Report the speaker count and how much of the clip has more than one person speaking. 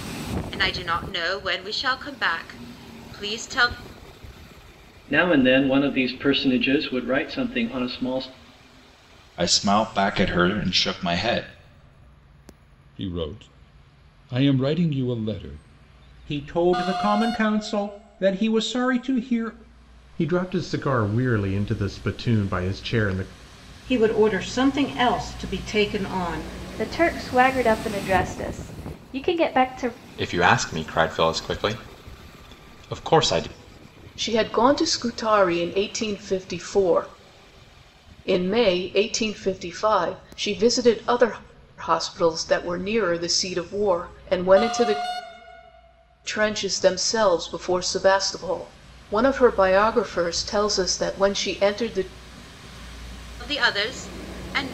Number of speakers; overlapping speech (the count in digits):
10, no overlap